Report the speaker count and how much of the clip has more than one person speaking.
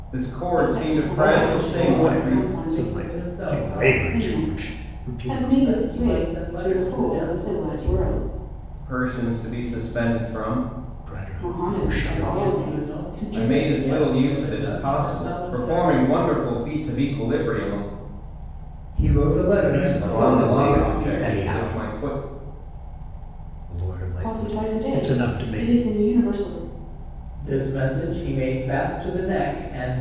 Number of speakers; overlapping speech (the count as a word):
four, about 53%